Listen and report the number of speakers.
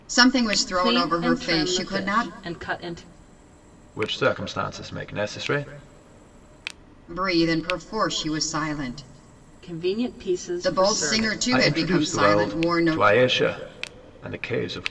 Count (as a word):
three